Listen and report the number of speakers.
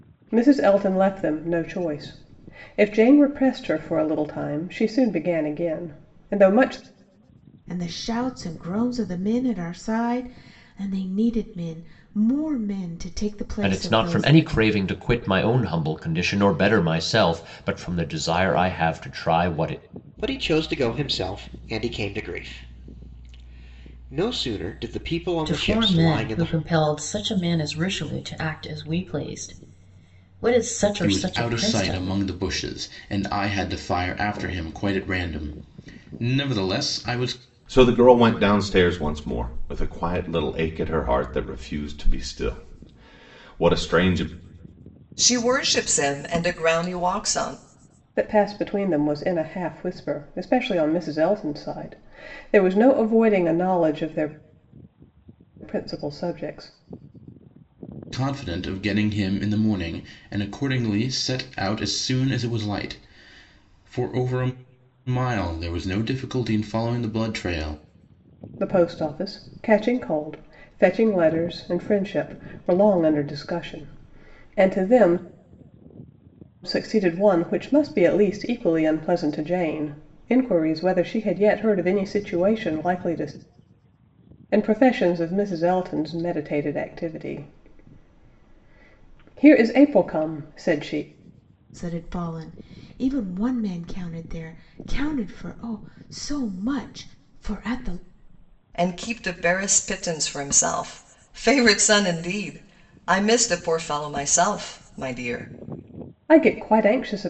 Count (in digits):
8